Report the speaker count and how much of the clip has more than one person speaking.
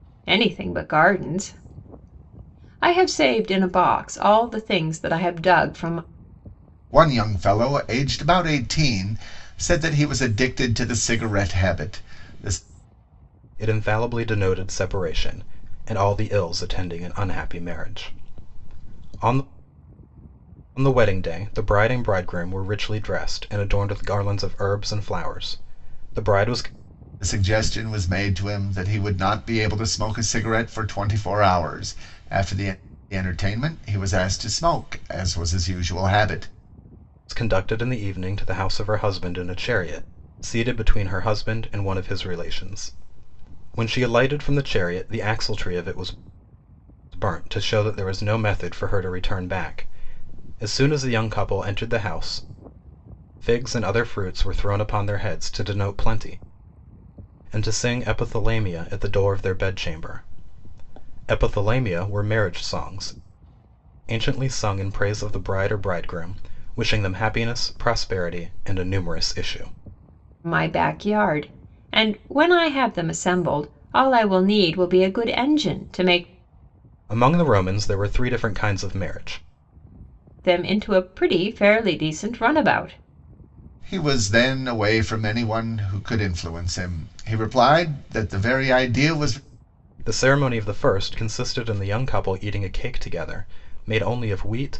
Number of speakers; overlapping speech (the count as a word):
three, no overlap